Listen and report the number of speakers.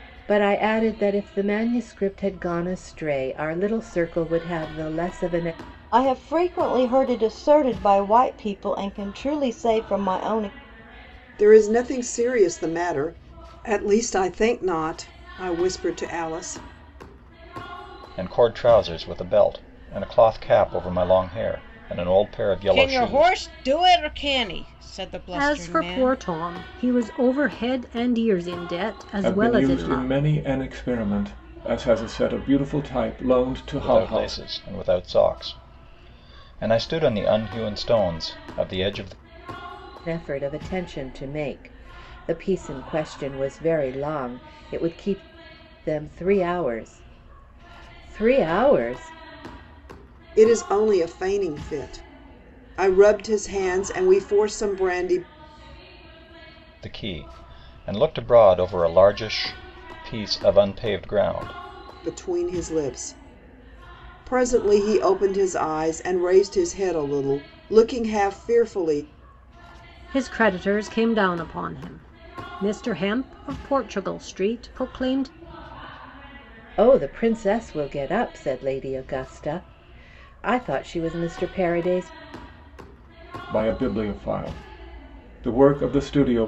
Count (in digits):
7